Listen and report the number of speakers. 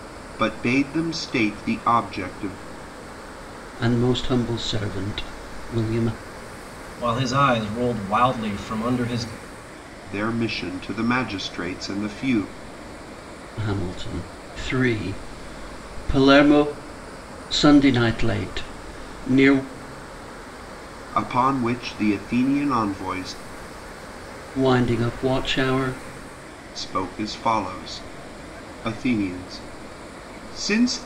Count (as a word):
three